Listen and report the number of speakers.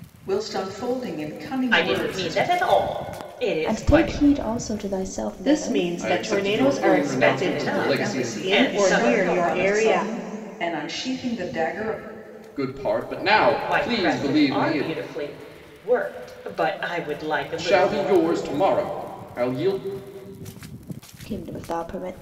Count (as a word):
five